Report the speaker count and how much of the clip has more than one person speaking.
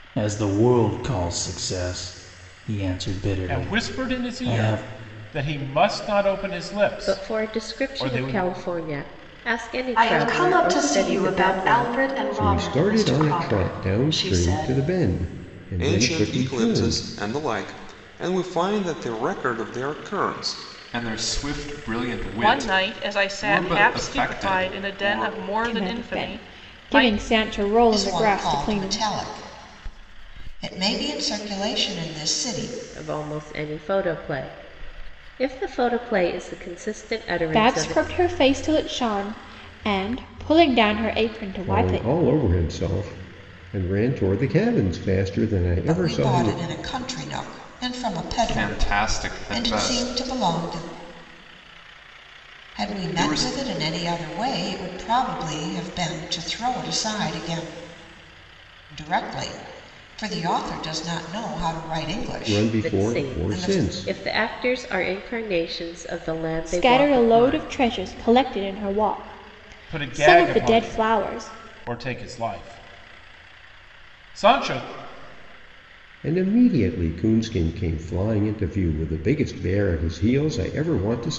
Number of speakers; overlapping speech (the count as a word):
ten, about 29%